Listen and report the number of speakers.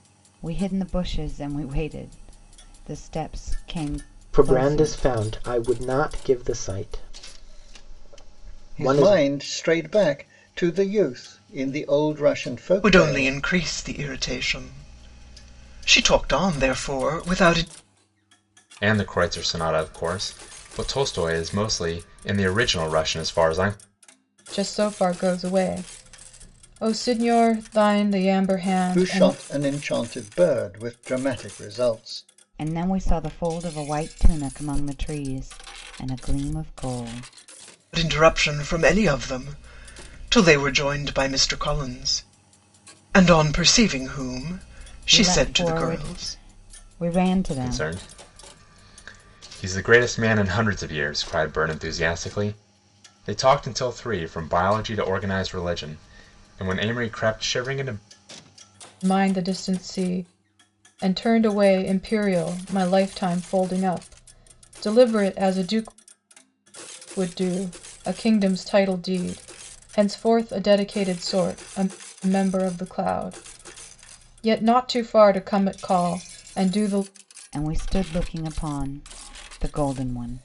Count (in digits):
6